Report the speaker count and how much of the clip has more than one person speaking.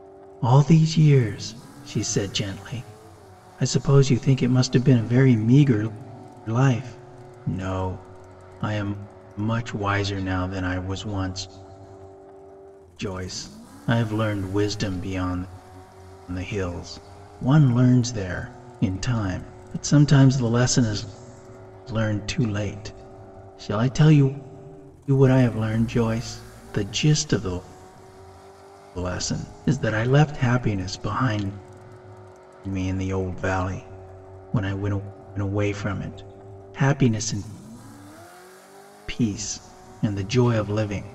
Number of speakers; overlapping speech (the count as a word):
one, no overlap